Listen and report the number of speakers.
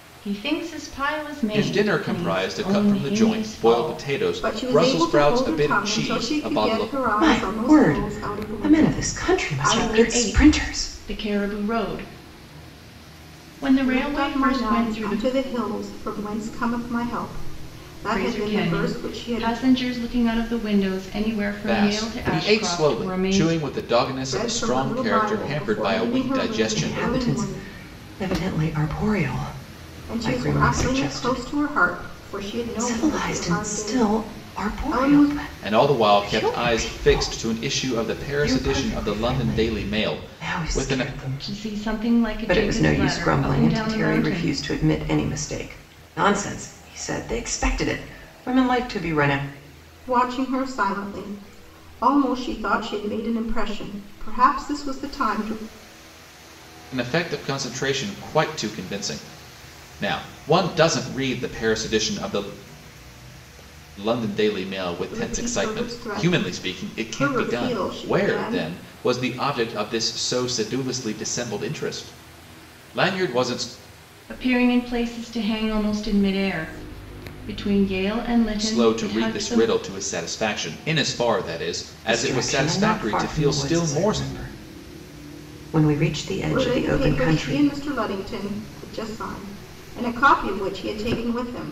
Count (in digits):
4